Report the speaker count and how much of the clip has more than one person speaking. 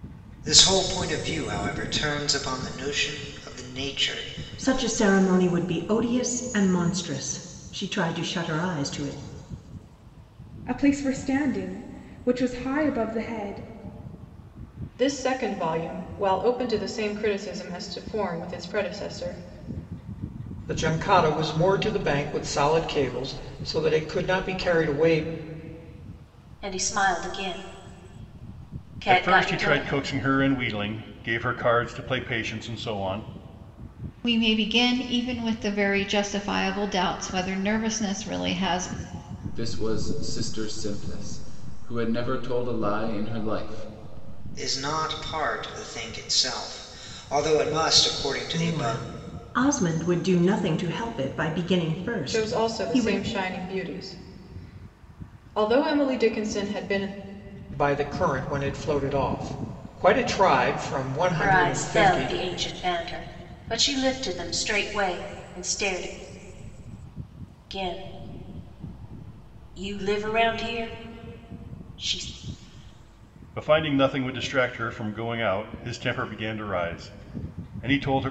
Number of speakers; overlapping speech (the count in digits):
9, about 5%